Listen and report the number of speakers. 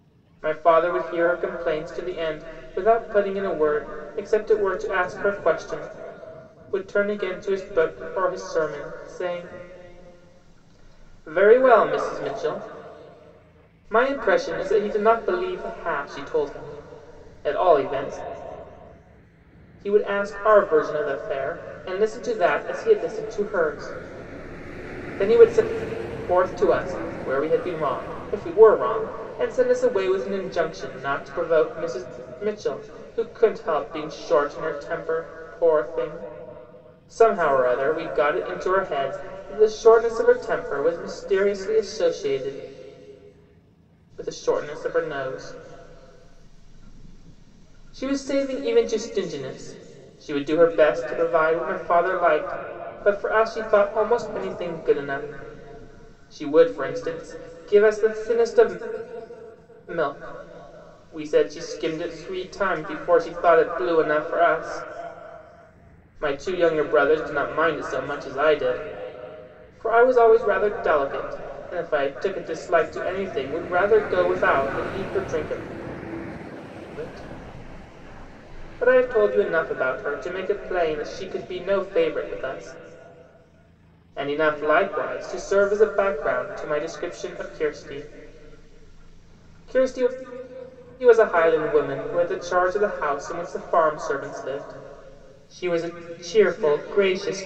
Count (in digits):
1